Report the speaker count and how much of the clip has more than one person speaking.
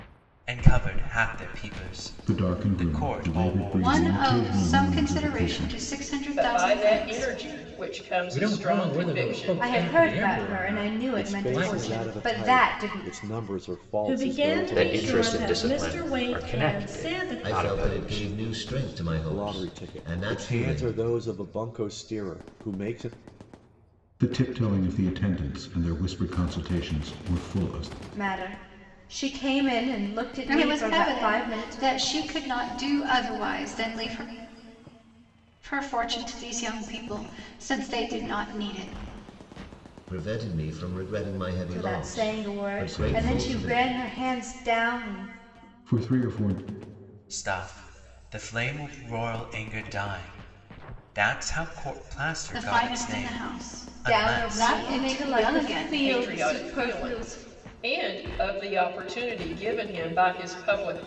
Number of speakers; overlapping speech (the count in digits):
10, about 42%